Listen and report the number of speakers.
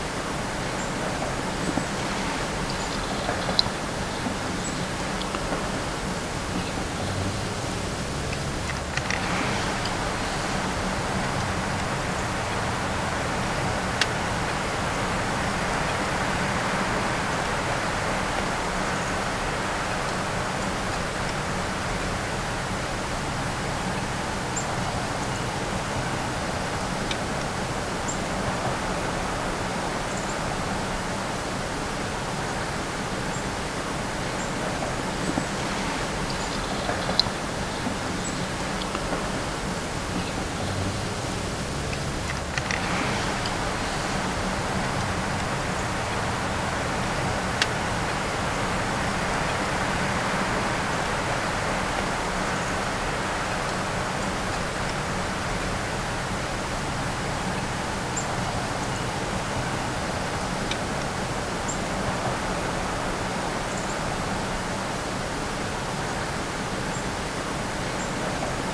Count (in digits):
0